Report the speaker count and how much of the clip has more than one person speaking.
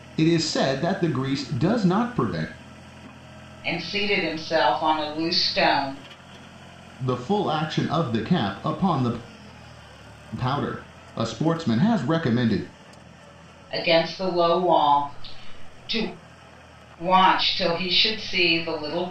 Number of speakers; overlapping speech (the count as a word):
two, no overlap